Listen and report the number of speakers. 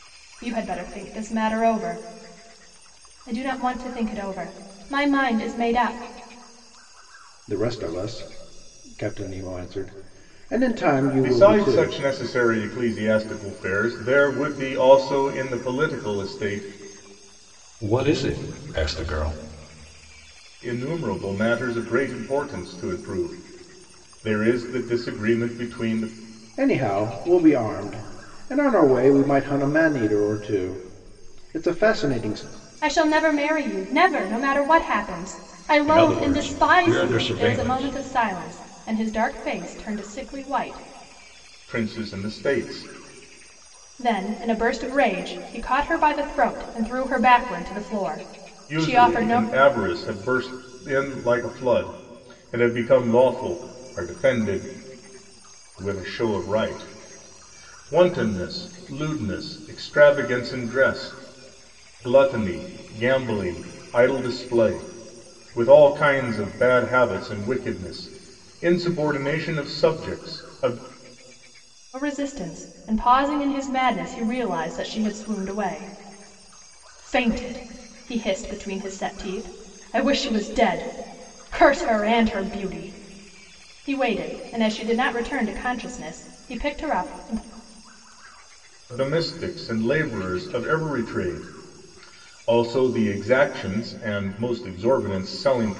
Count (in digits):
4